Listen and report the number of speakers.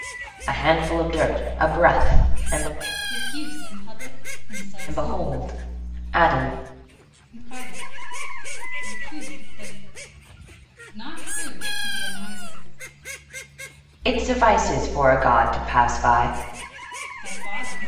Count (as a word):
two